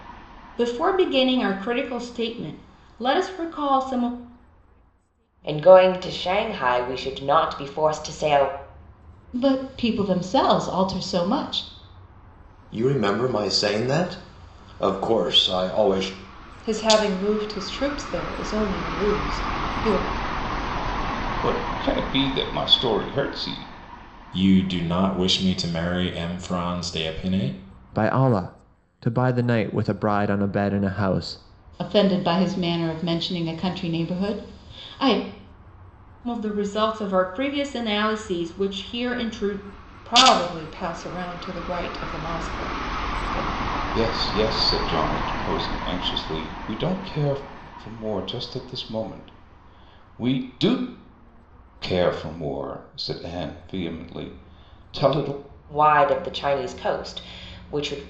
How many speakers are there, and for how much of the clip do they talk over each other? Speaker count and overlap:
eight, no overlap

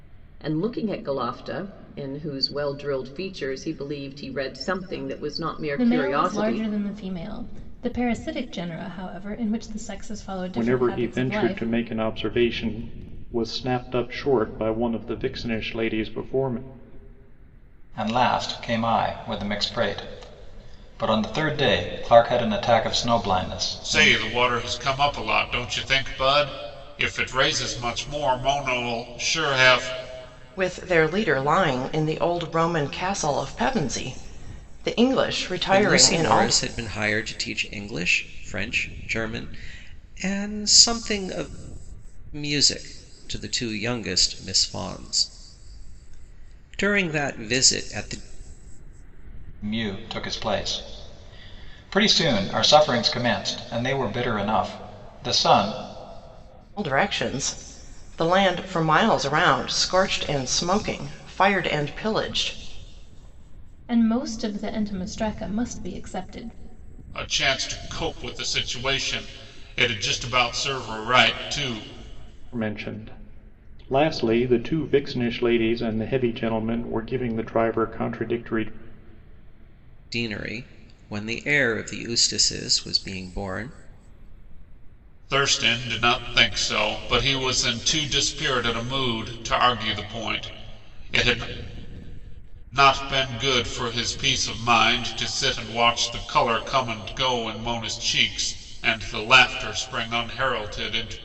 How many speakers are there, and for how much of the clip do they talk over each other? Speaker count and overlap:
seven, about 3%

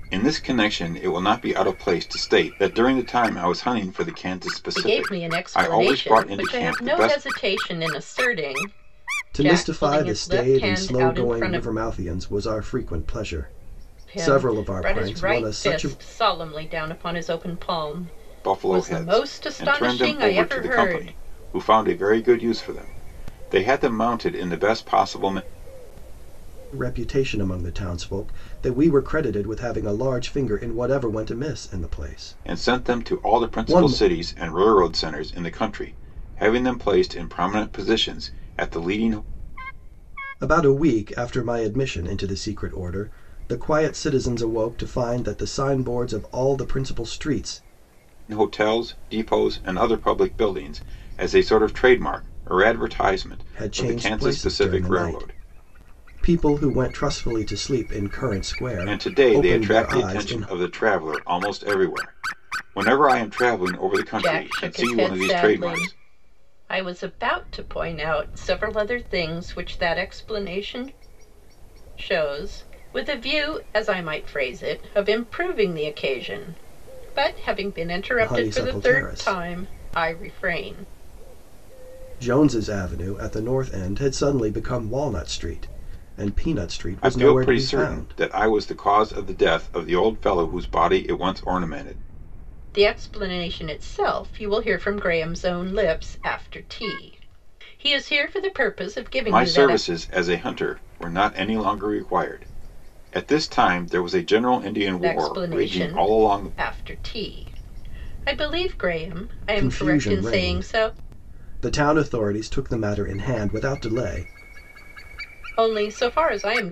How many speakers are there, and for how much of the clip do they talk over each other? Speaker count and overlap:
three, about 19%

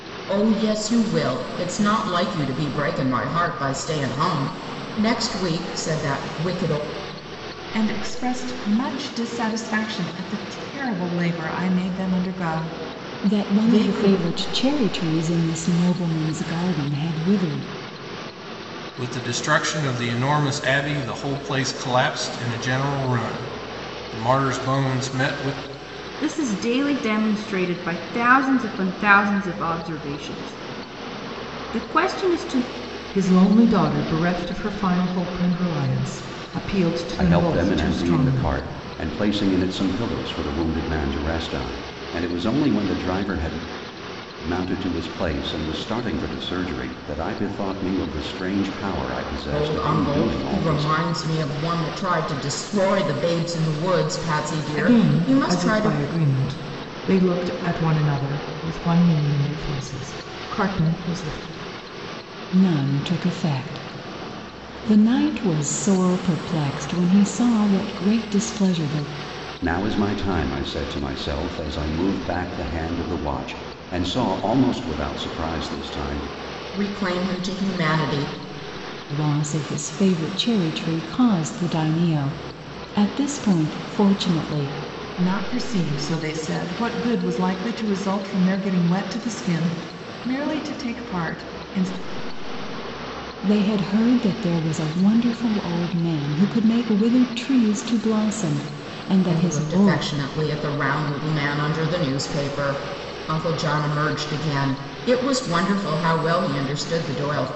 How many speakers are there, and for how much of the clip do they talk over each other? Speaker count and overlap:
seven, about 6%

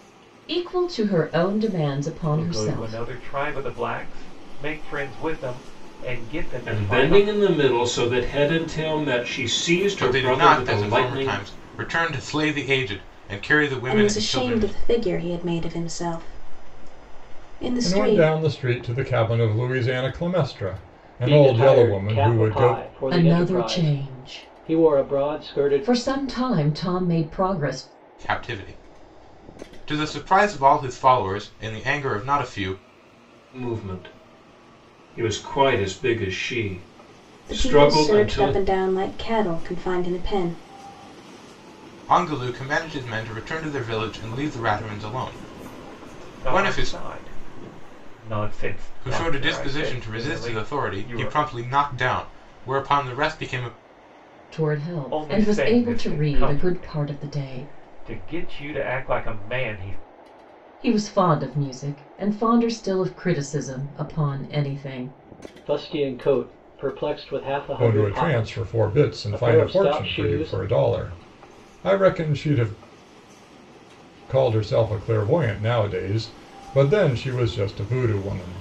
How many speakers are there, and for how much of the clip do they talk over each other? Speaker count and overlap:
seven, about 23%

